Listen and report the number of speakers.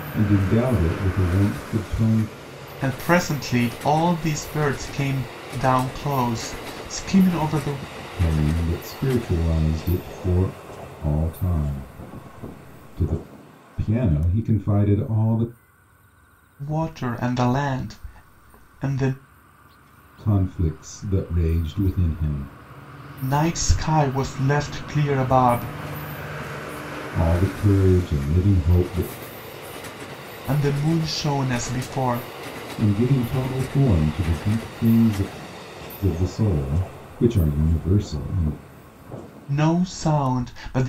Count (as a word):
two